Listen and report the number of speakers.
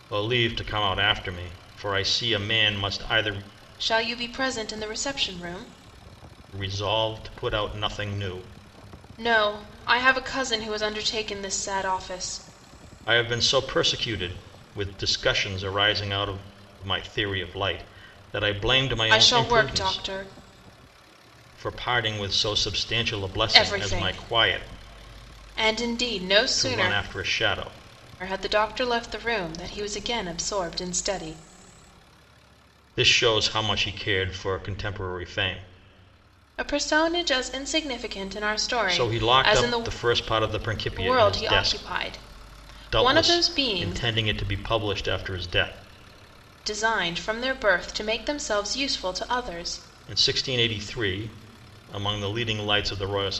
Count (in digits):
2